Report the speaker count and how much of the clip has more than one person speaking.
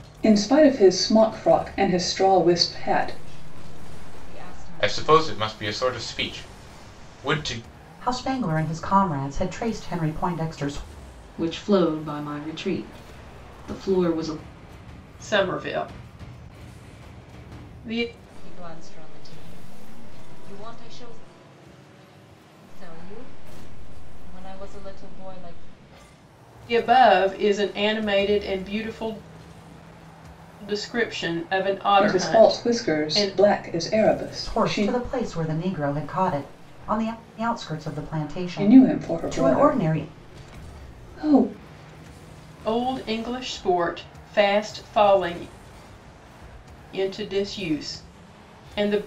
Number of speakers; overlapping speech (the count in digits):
6, about 9%